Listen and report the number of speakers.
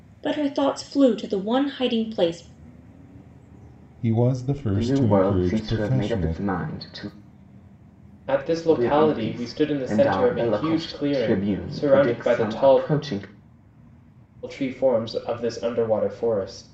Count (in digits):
4